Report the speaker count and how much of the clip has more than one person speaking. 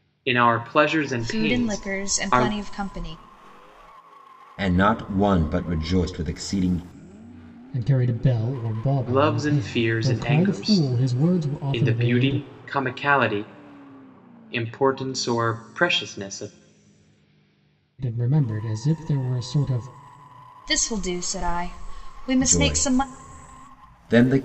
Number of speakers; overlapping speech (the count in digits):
4, about 18%